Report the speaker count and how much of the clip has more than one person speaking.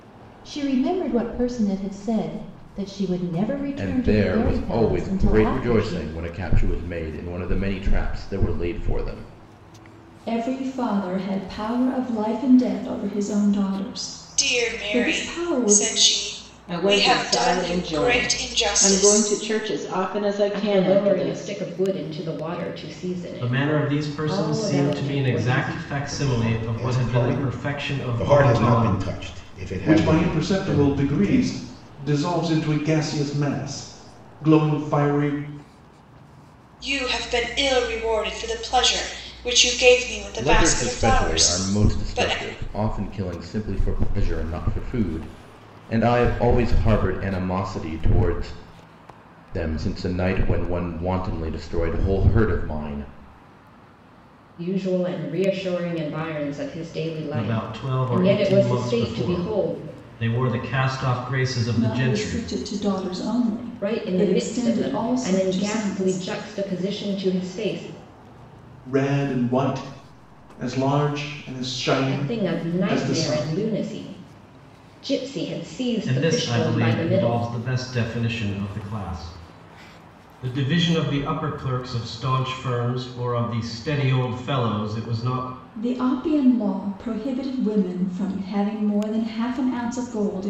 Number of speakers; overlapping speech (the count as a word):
nine, about 28%